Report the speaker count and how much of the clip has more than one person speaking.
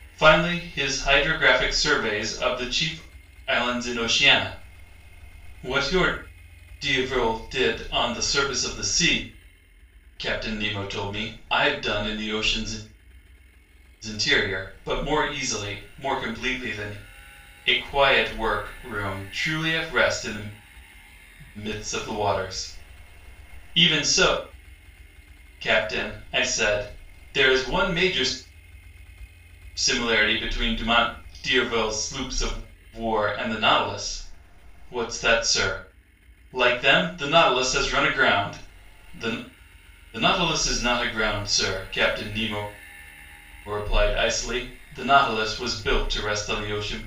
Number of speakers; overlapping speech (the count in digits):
1, no overlap